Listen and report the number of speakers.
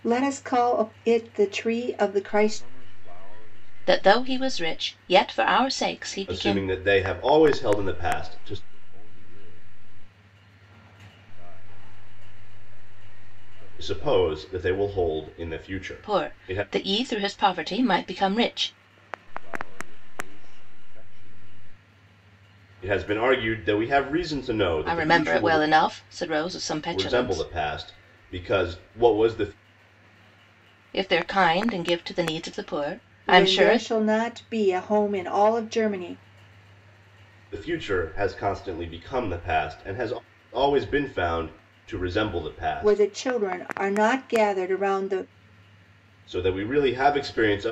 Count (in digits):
4